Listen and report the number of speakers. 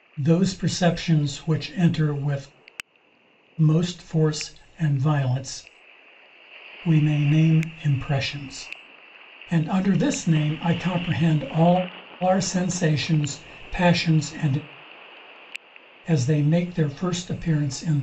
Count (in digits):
1